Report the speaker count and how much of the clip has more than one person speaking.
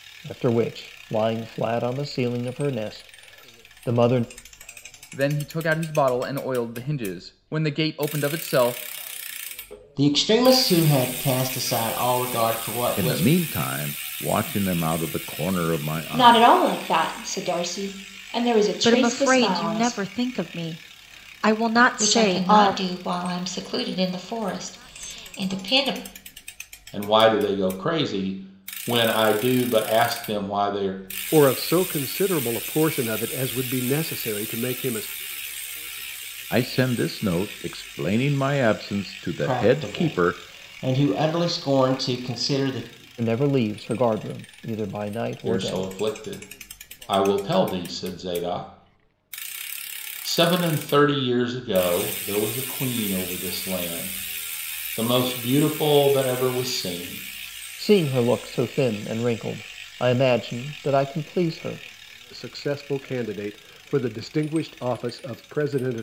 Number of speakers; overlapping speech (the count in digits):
9, about 7%